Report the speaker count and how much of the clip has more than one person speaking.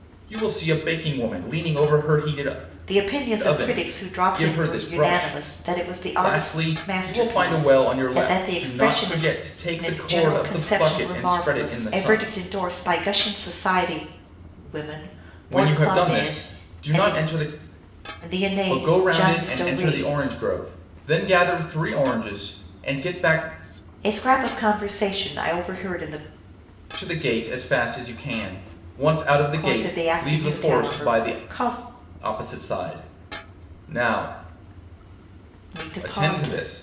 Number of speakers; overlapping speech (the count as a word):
two, about 36%